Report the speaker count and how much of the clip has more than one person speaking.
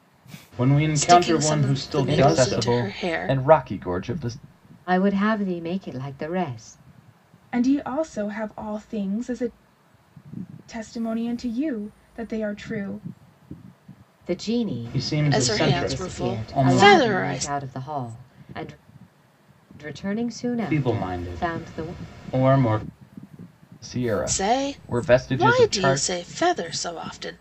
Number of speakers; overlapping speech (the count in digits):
5, about 30%